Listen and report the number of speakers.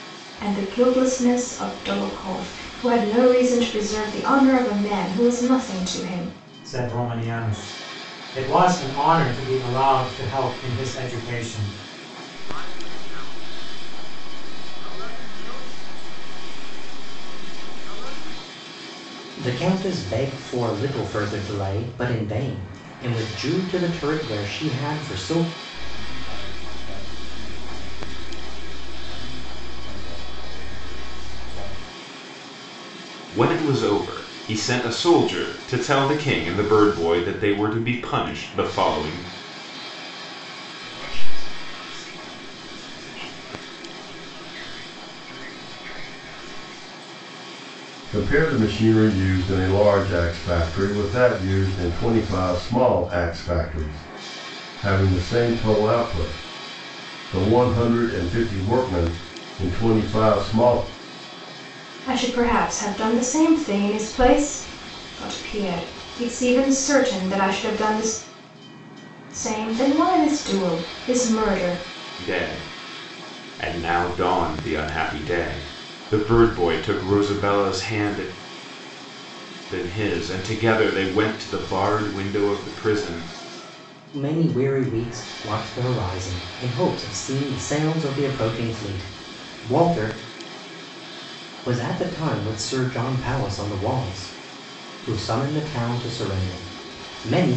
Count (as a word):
eight